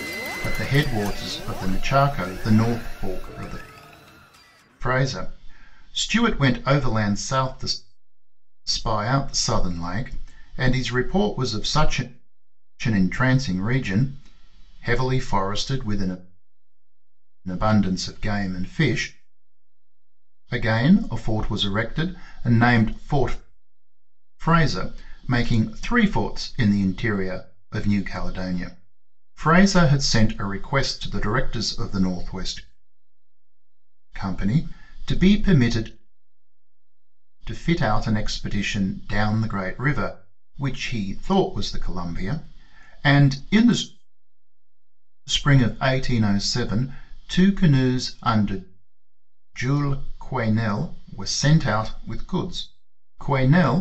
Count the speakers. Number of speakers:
1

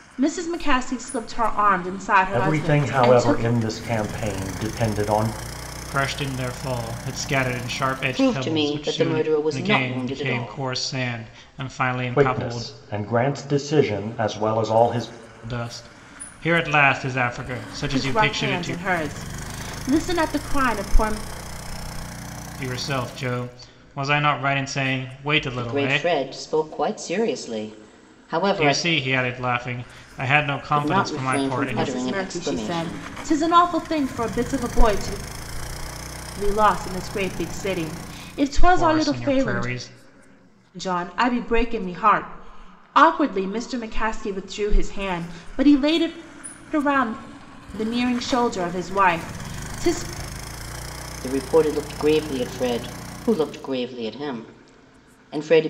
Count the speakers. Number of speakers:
4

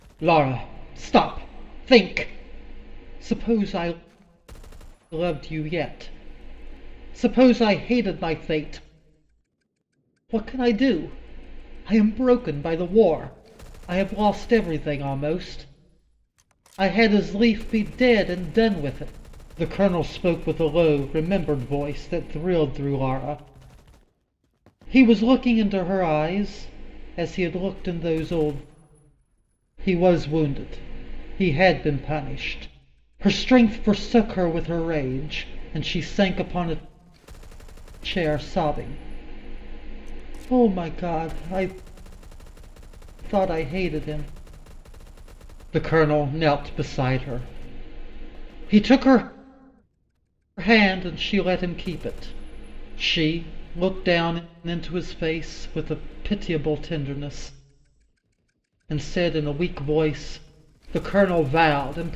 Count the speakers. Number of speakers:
1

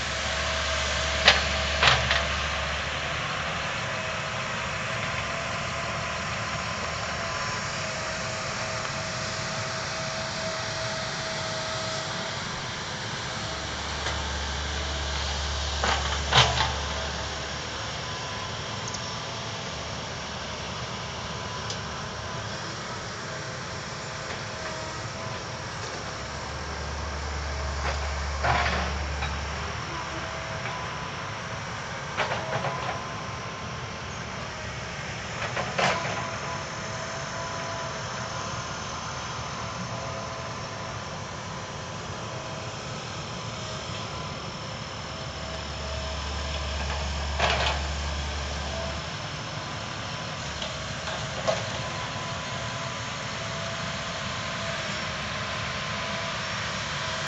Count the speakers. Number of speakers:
0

